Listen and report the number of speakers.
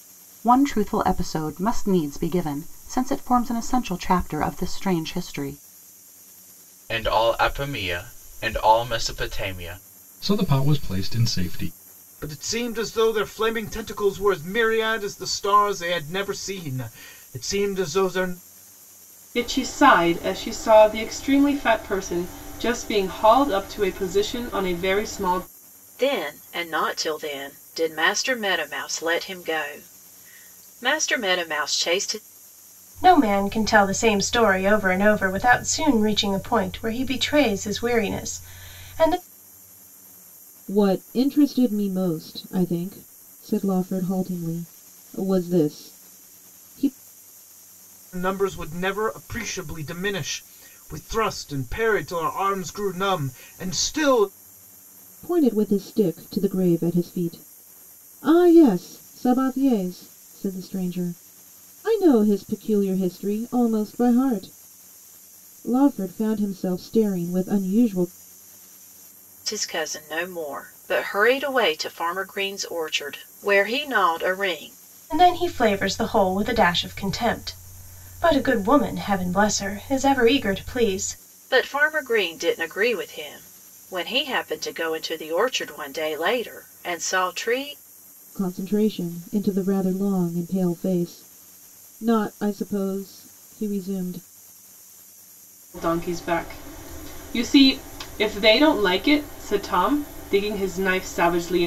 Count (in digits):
8